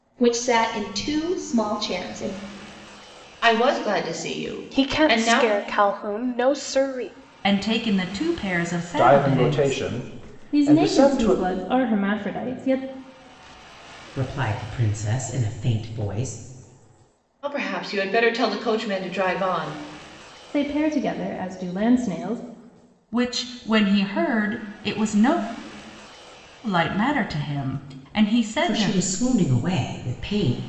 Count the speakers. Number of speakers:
seven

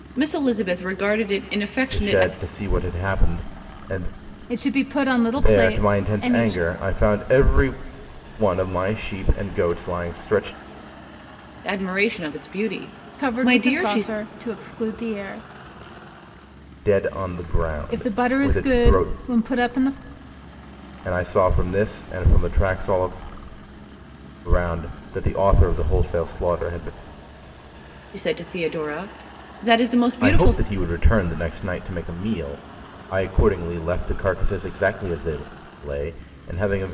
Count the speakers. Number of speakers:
three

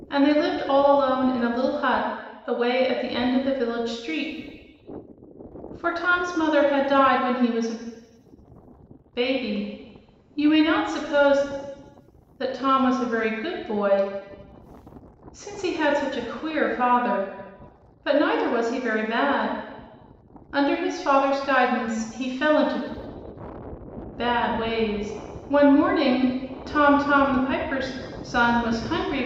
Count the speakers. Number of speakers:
one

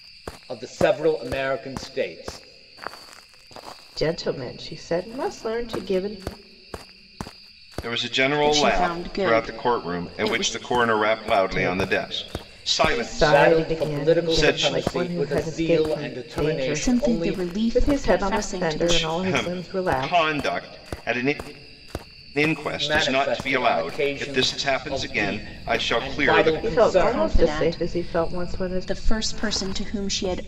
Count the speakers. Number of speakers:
four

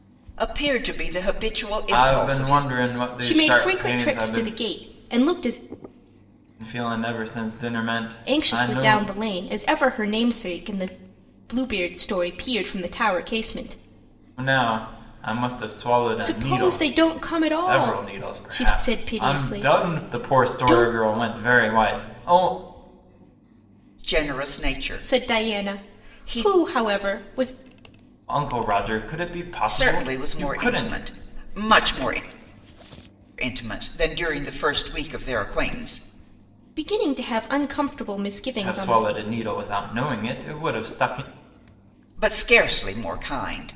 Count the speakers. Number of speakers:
three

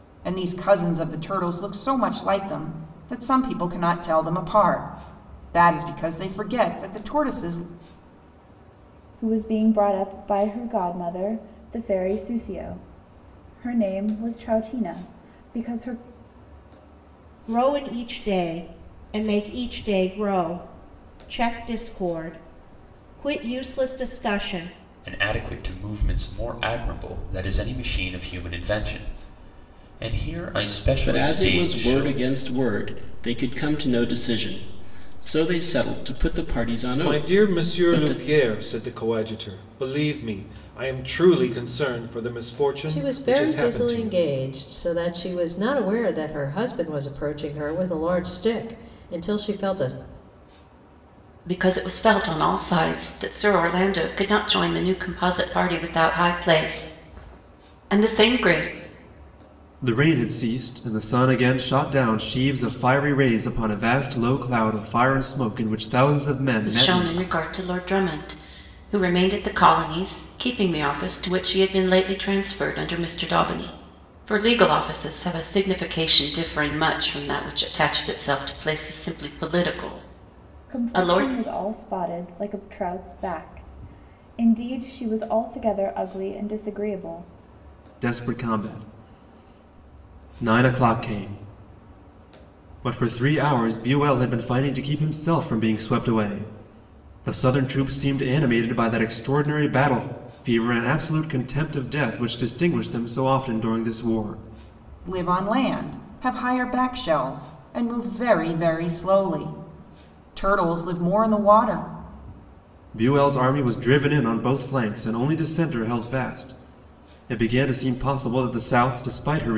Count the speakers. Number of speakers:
nine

